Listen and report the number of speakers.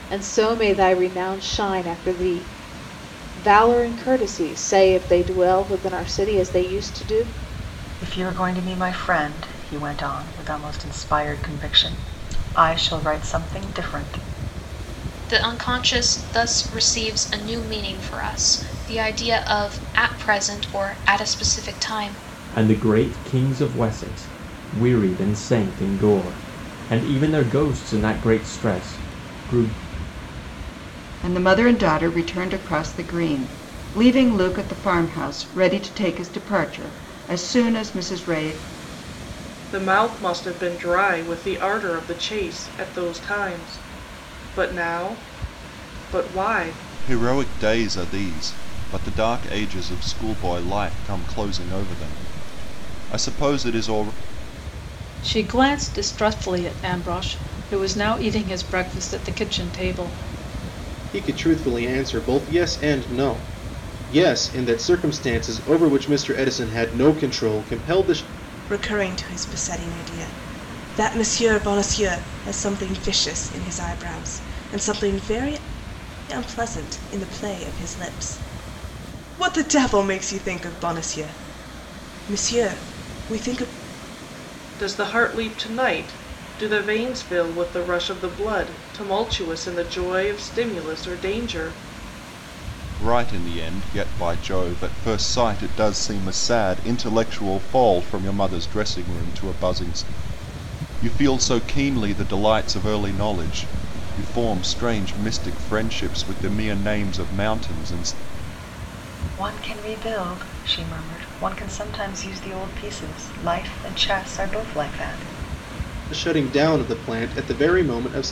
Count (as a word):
ten